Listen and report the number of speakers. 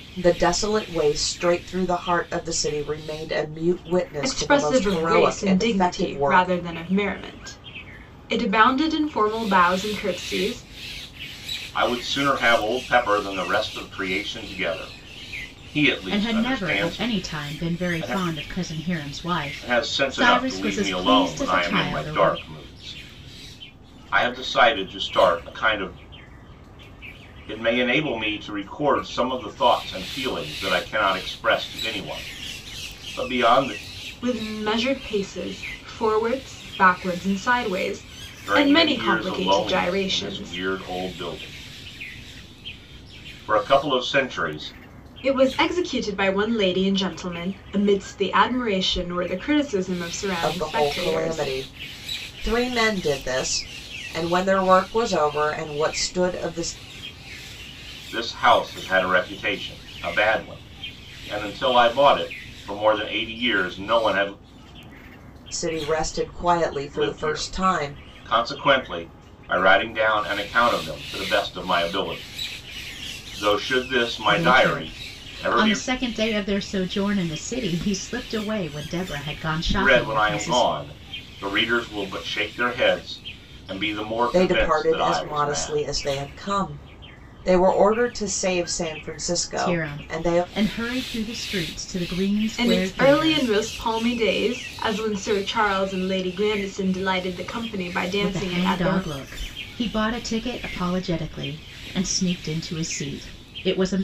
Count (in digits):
4